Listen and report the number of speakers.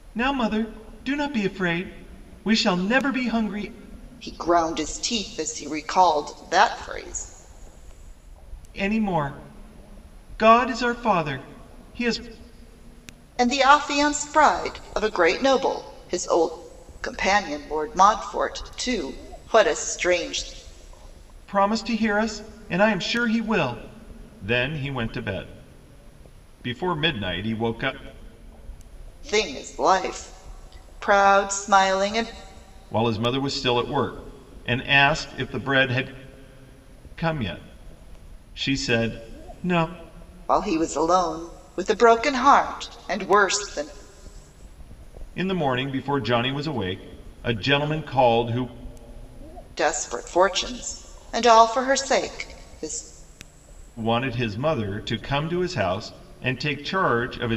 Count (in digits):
2